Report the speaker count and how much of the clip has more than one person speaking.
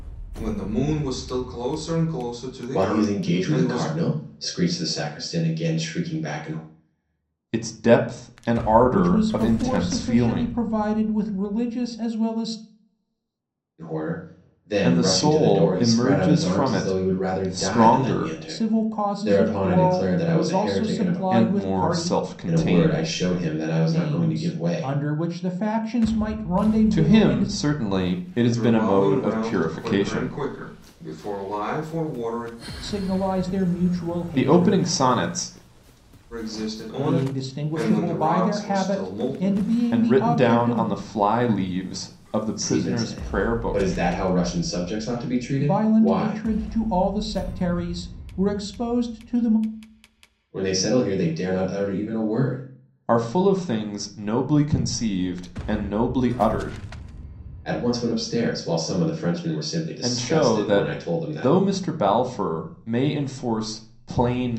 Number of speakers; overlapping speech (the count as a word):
four, about 35%